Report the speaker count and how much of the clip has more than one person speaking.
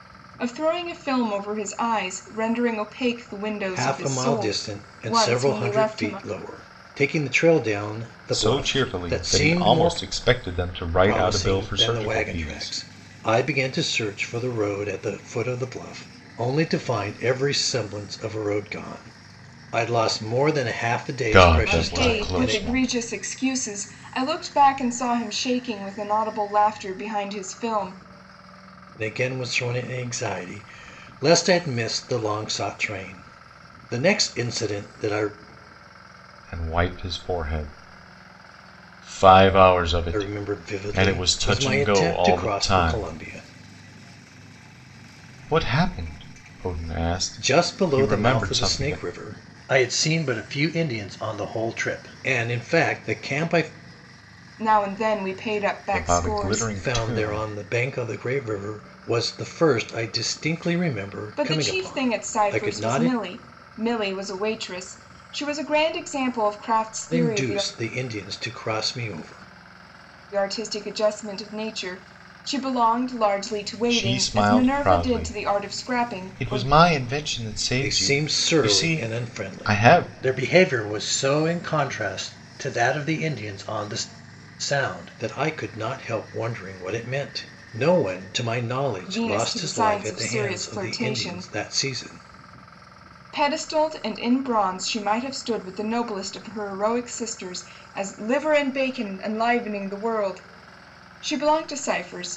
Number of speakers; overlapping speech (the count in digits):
3, about 24%